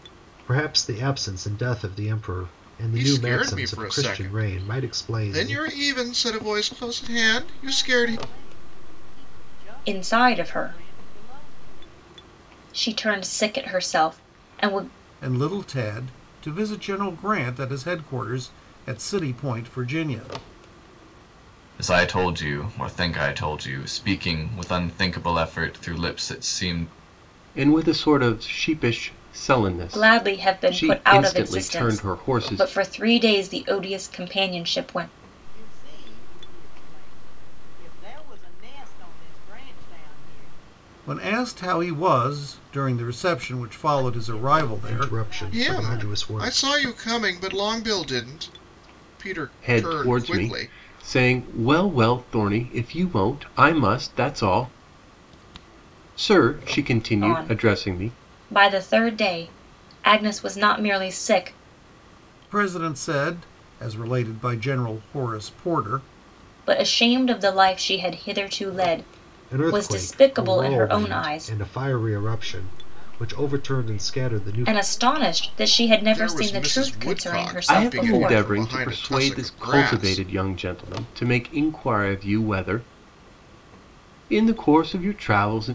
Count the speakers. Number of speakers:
7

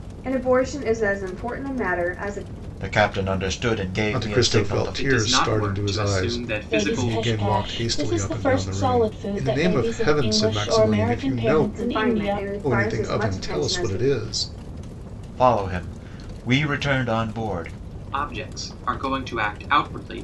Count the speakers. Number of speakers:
5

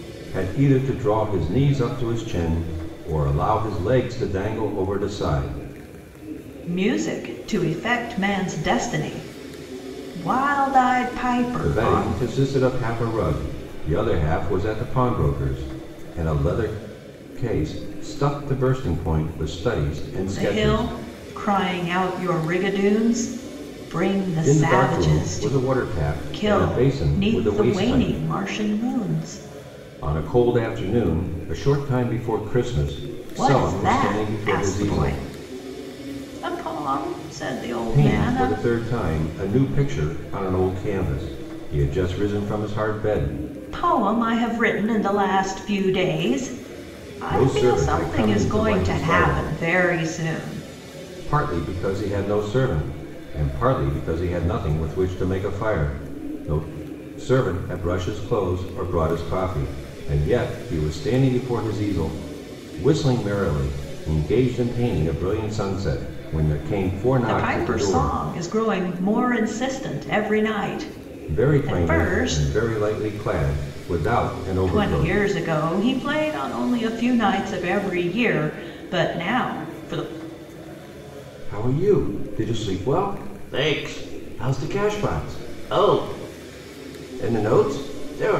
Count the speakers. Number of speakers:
2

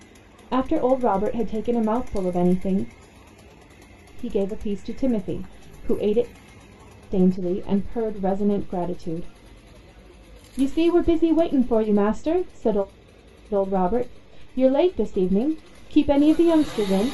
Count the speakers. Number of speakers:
1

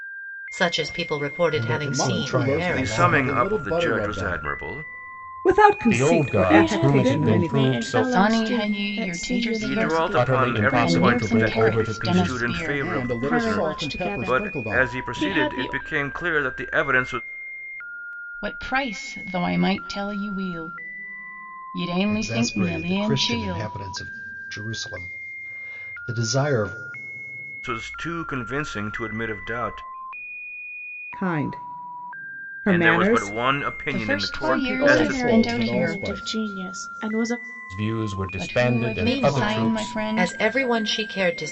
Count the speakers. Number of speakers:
8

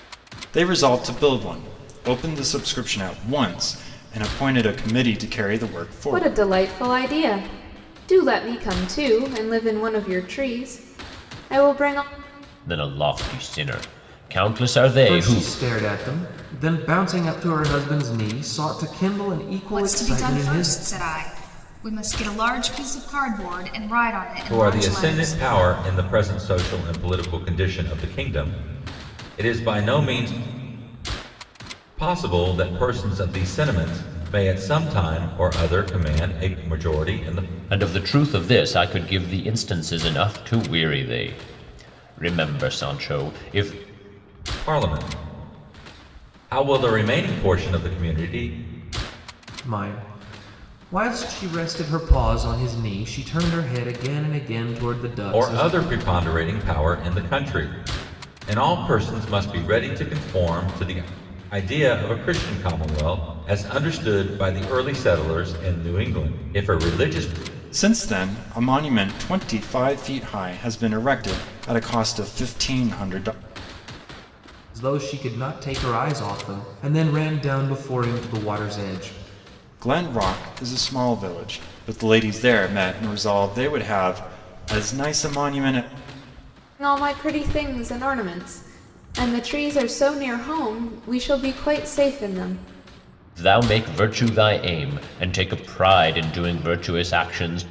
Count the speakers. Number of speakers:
6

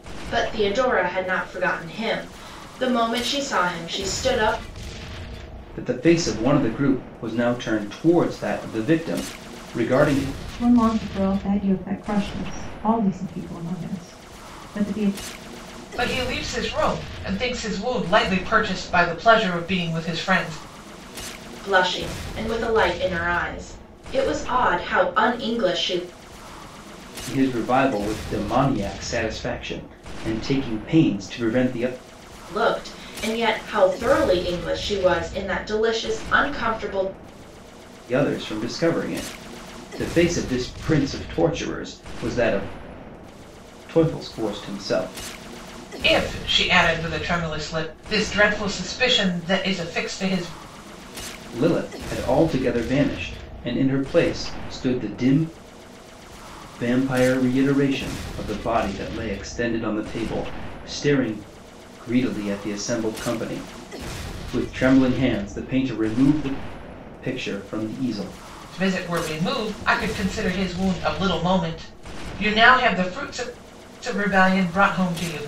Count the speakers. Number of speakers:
4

